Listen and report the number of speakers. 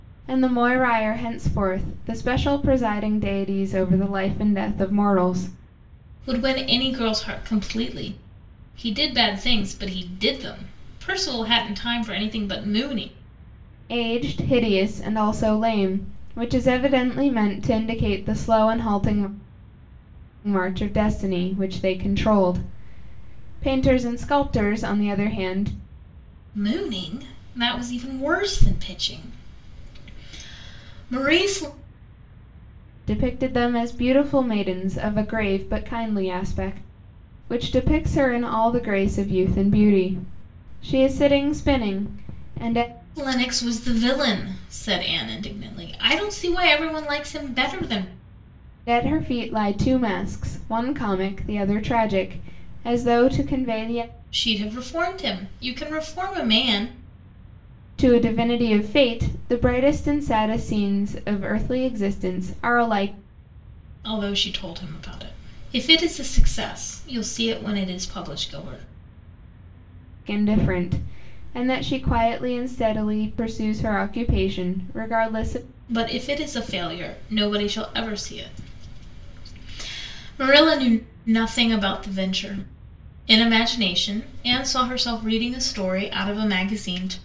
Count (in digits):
2